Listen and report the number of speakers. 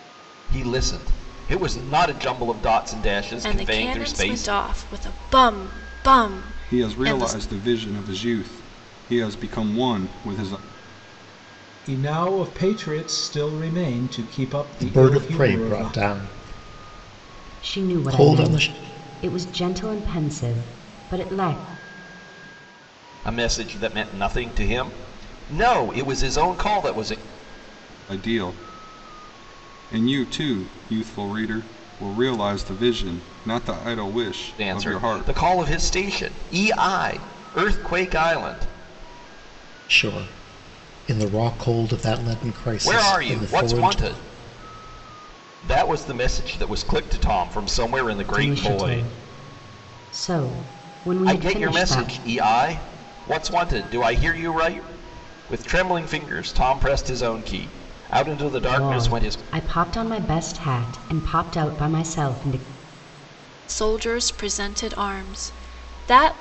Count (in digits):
6